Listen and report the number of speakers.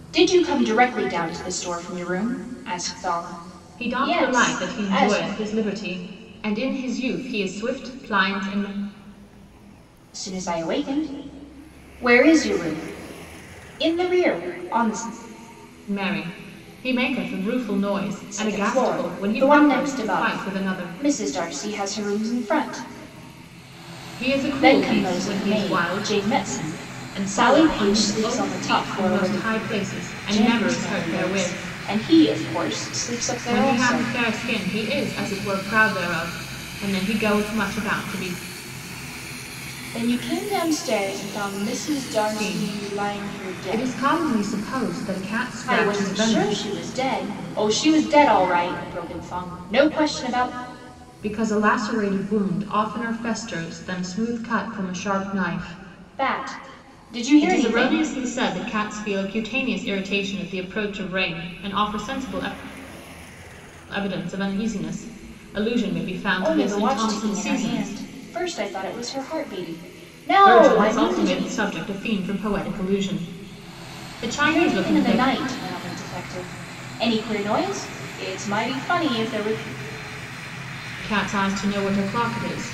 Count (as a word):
two